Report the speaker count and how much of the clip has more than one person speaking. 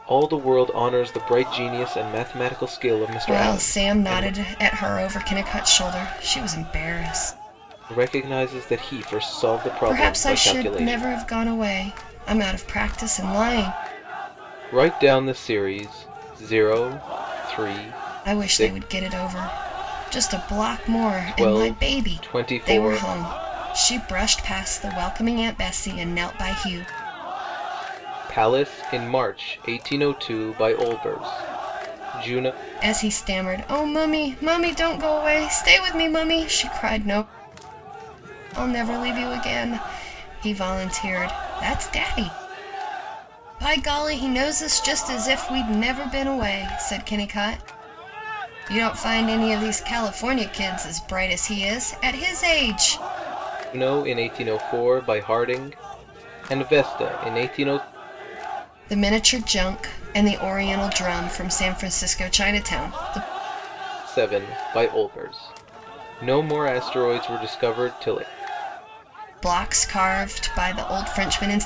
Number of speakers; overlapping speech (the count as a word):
two, about 6%